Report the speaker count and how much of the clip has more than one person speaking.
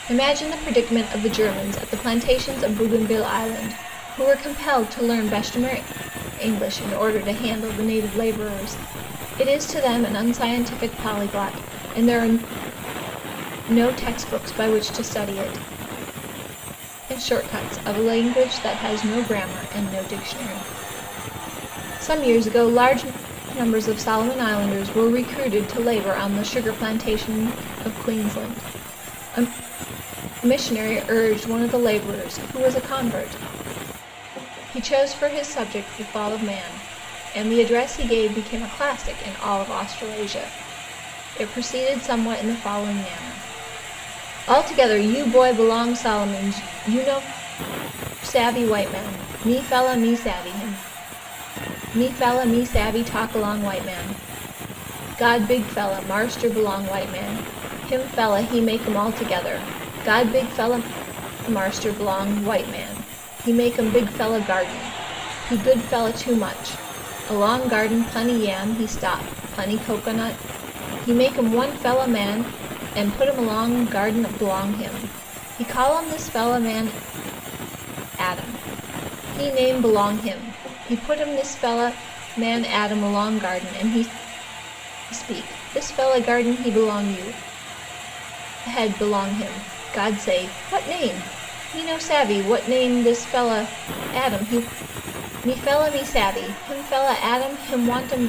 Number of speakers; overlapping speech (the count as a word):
one, no overlap